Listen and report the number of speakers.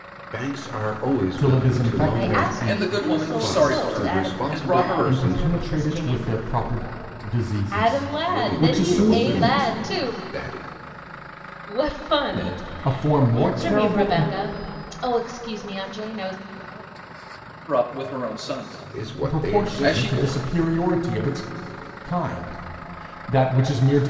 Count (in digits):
4